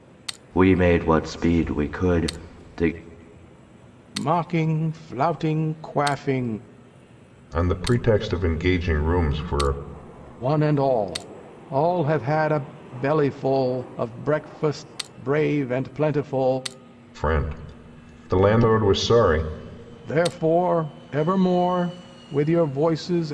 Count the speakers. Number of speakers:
three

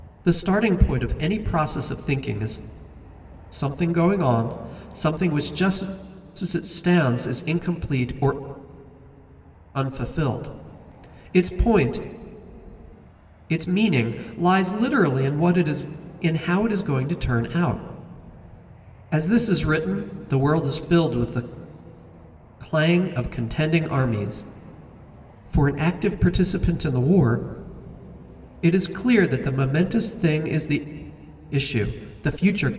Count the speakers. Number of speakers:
one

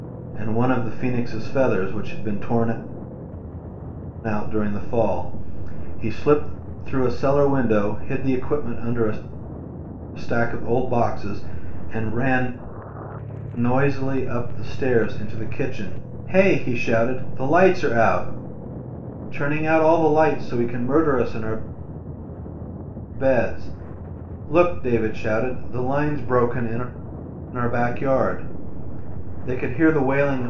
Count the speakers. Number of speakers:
one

